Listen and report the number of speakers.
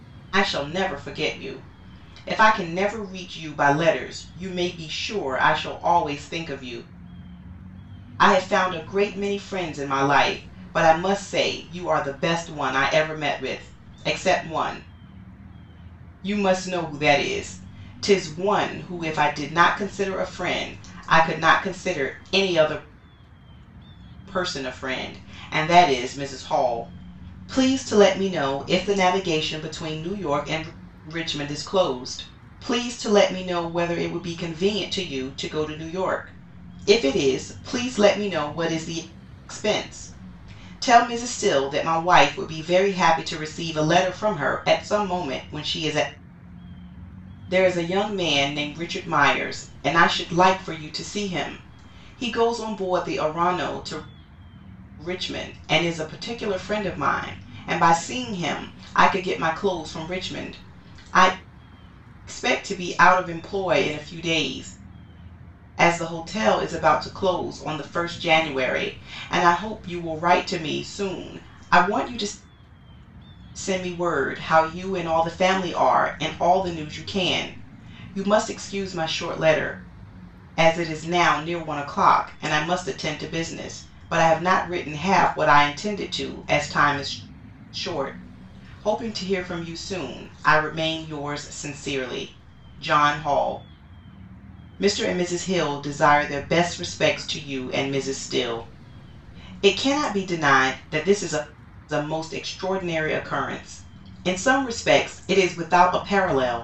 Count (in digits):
1